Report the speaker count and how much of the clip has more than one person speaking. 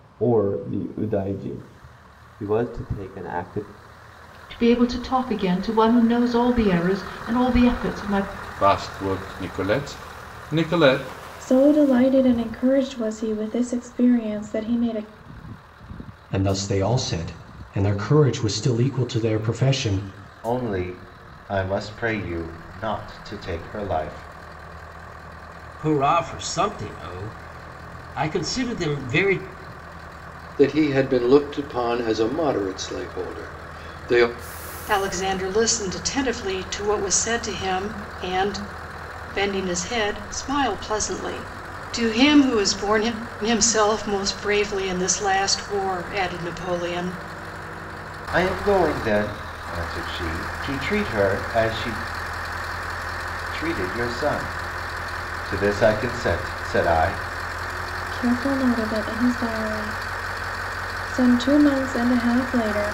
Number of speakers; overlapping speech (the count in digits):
9, no overlap